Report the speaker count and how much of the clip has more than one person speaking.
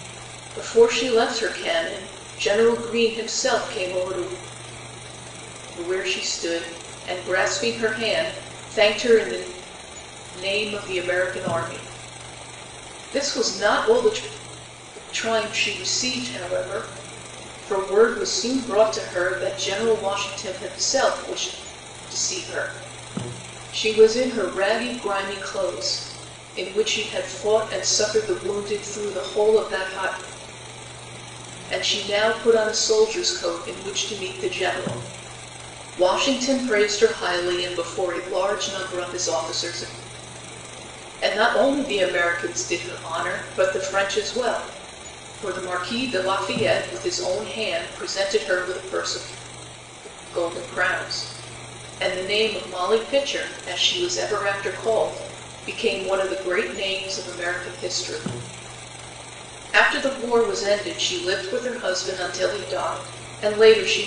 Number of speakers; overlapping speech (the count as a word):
one, no overlap